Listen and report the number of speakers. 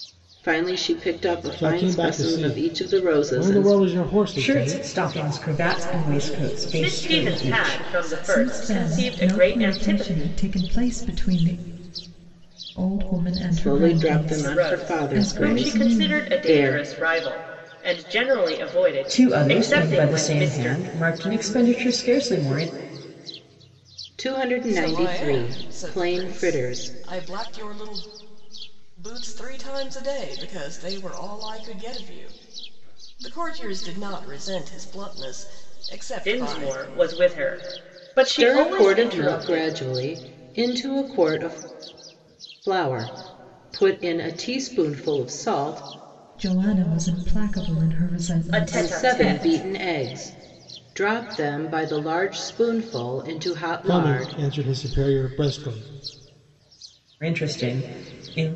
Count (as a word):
six